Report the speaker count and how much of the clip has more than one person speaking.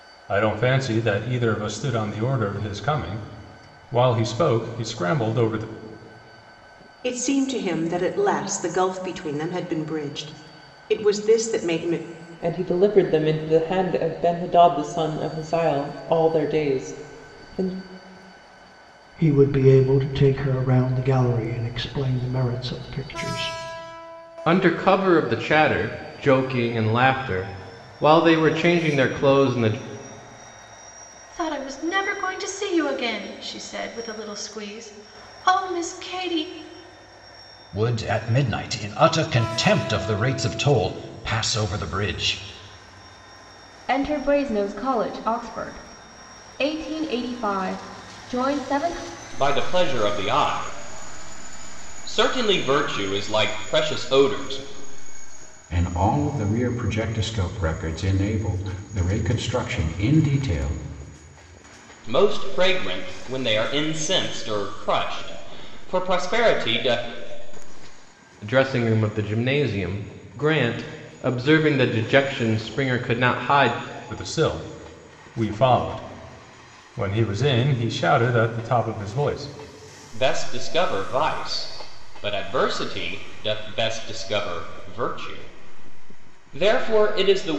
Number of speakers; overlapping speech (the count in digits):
10, no overlap